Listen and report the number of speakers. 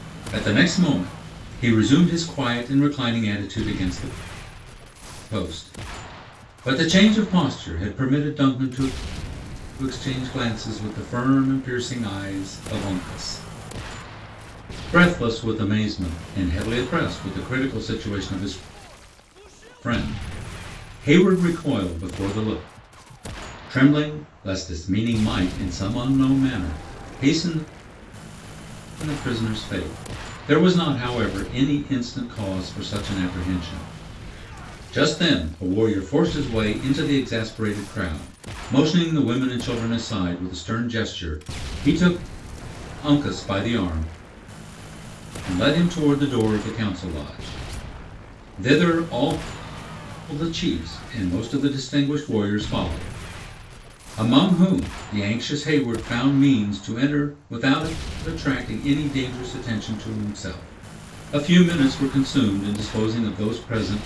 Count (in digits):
1